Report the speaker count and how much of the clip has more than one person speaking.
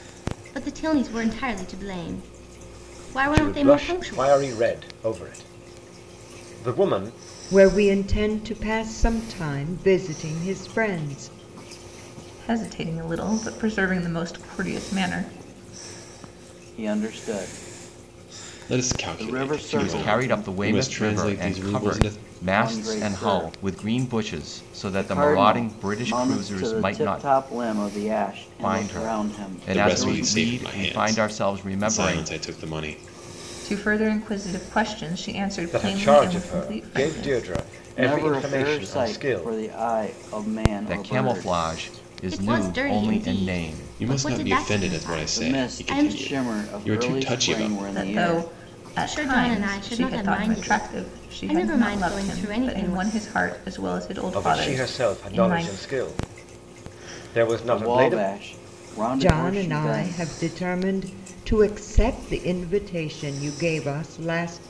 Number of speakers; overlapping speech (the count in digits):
7, about 48%